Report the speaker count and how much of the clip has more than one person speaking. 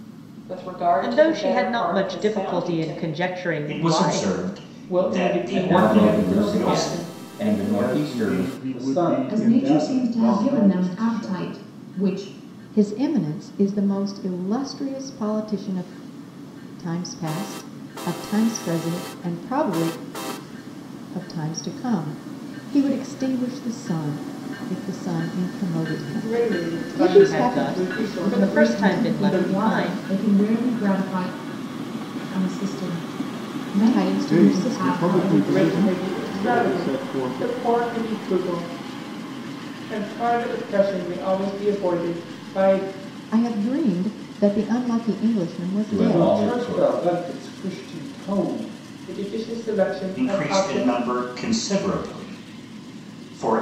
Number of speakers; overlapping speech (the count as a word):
nine, about 36%